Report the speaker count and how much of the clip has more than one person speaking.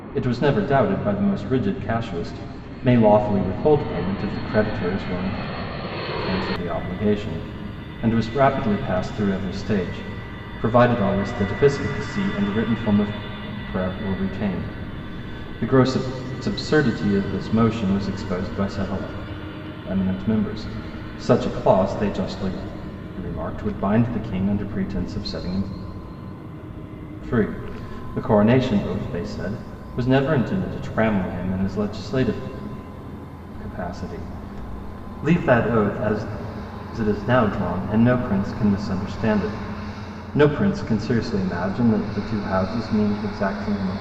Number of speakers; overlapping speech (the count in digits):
1, no overlap